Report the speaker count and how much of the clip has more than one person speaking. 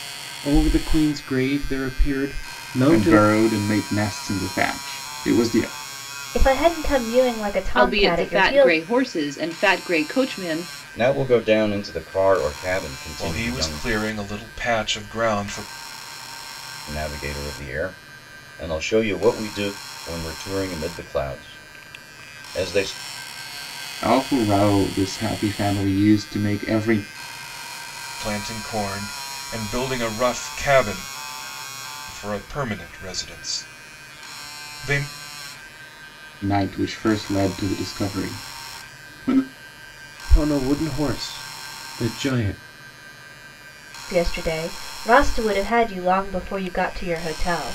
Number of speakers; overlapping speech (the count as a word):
six, about 5%